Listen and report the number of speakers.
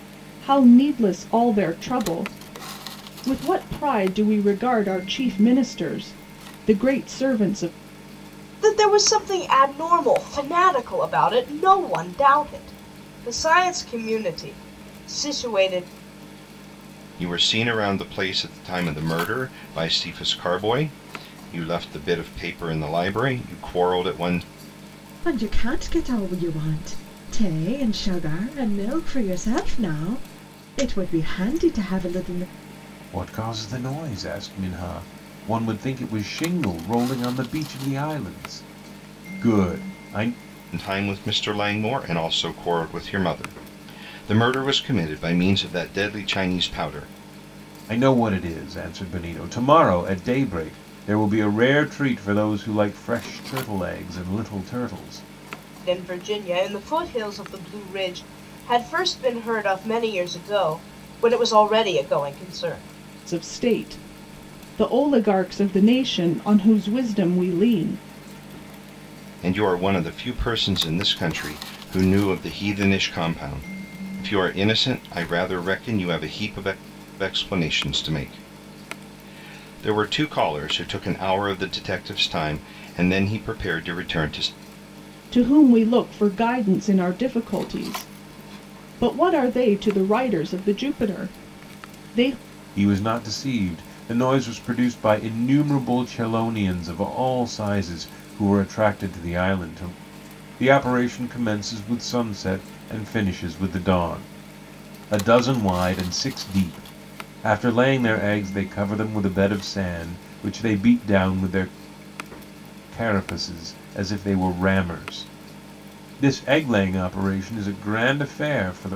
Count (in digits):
5